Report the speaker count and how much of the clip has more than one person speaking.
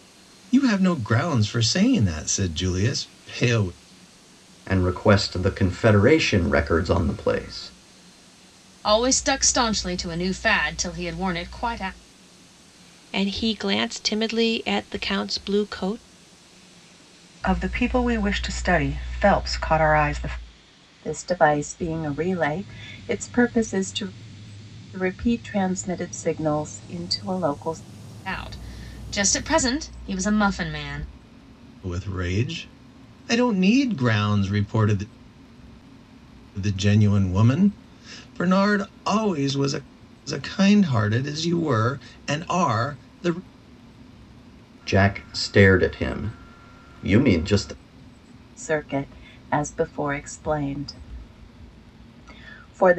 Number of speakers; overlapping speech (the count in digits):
6, no overlap